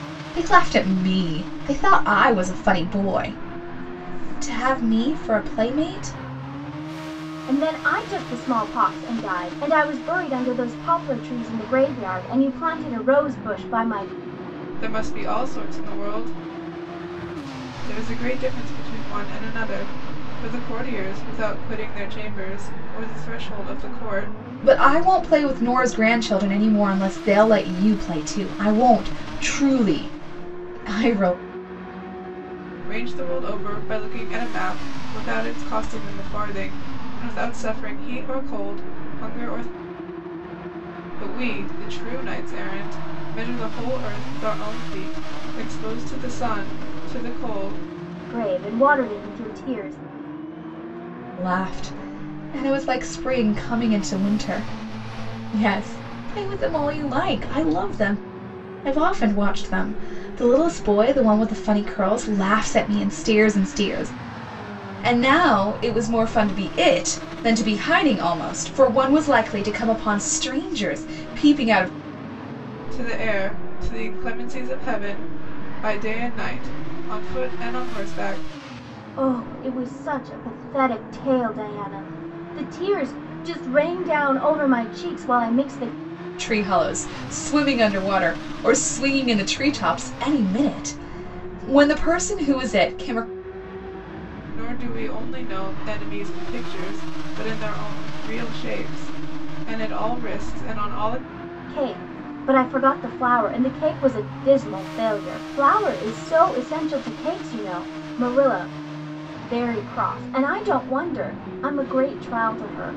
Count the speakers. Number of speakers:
3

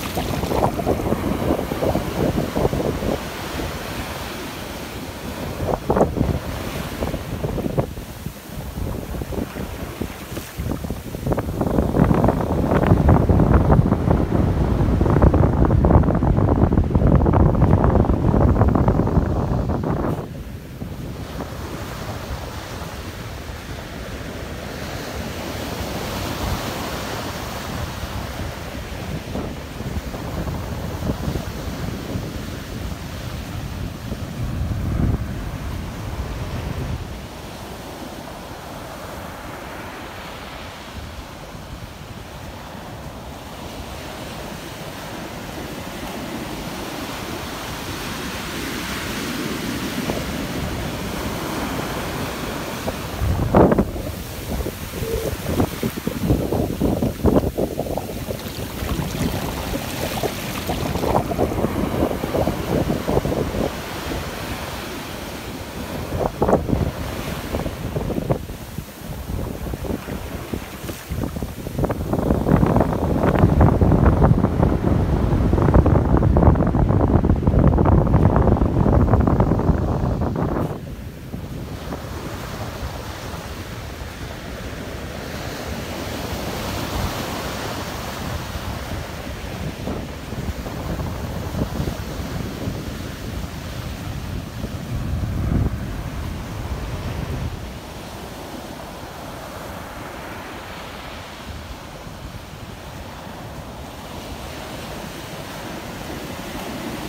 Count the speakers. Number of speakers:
0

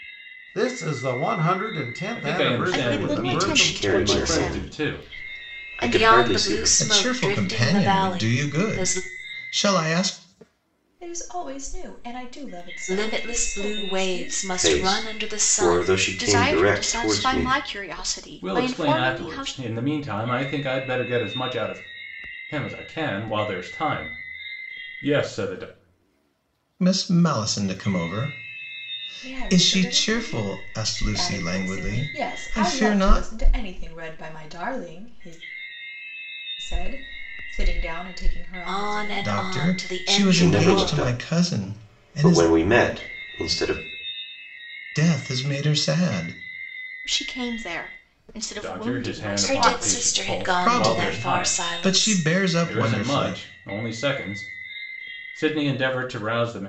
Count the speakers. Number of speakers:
7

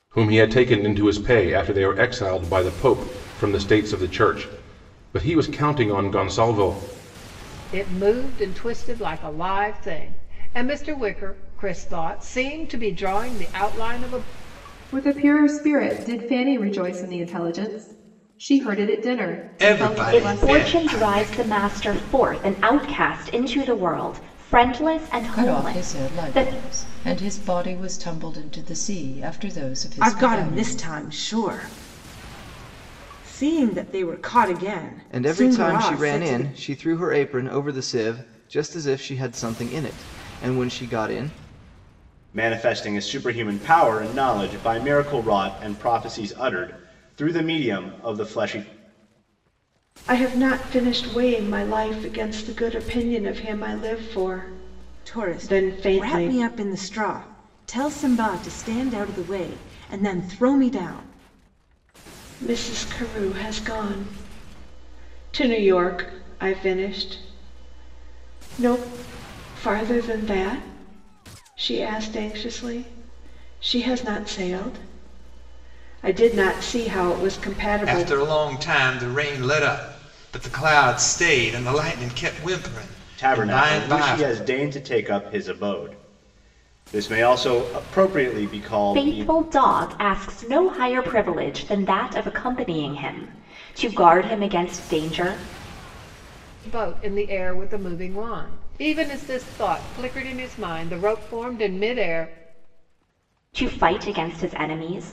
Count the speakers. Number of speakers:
10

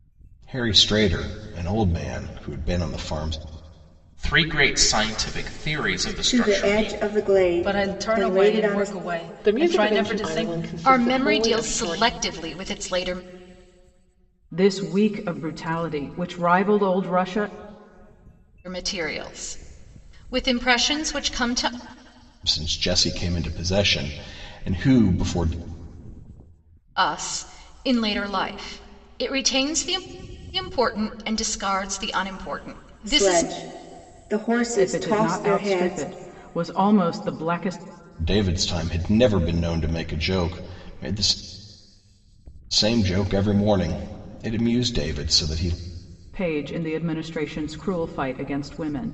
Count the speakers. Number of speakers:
7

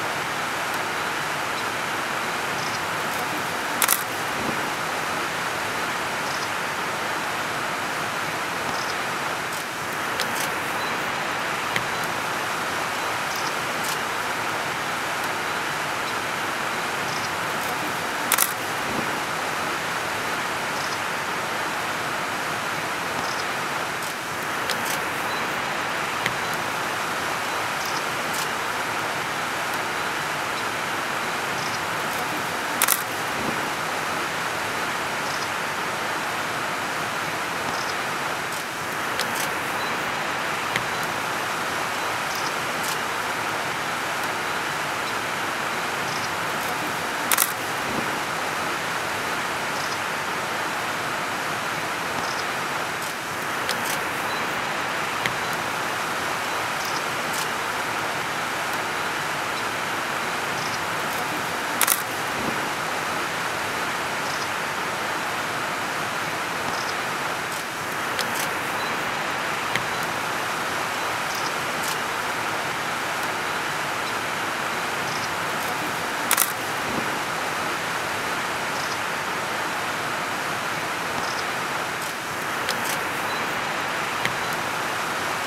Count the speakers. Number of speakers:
0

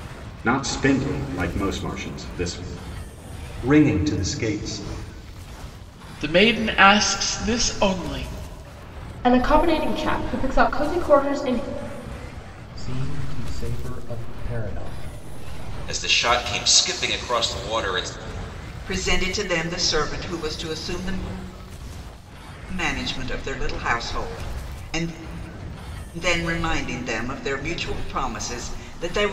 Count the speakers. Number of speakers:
7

